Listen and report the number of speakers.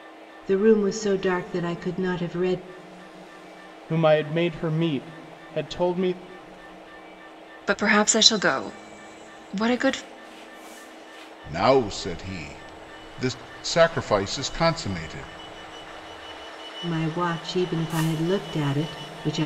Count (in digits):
4